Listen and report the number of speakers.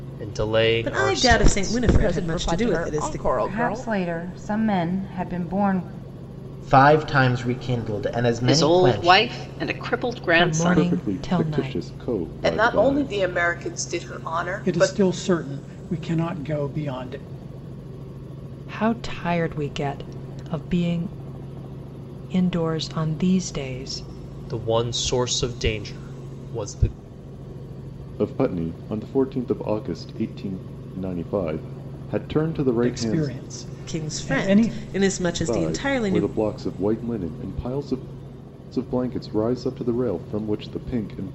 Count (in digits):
10